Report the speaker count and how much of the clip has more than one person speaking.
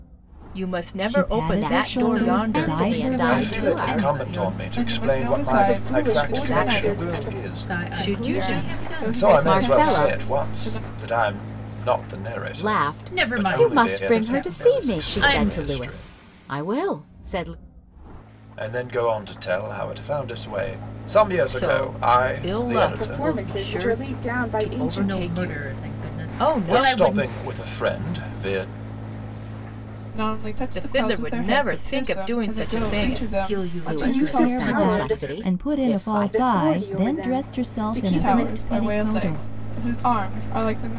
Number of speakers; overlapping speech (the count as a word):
seven, about 67%